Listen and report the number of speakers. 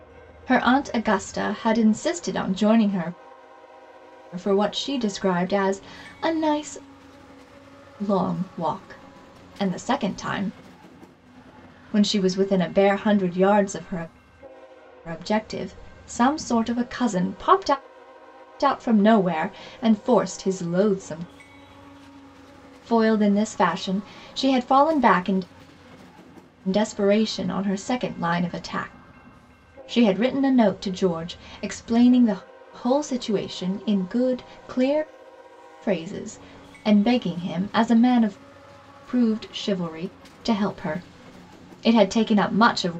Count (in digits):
1